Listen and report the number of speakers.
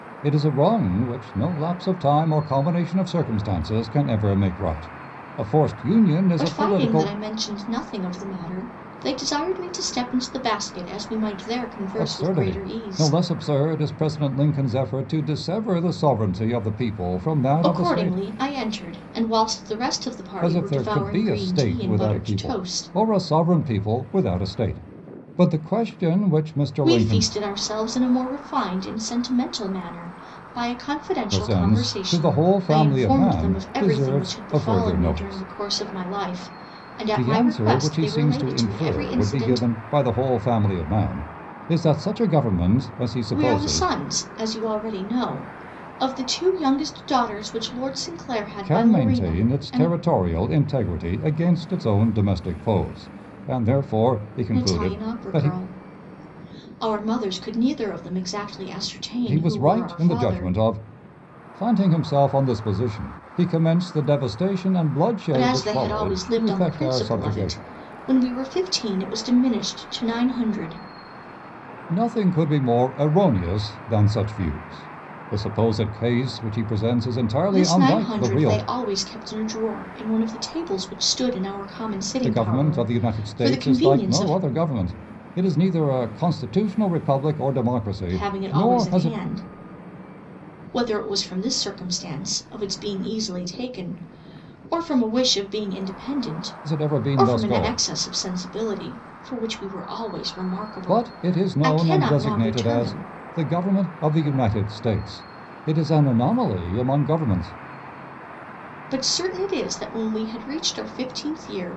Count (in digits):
2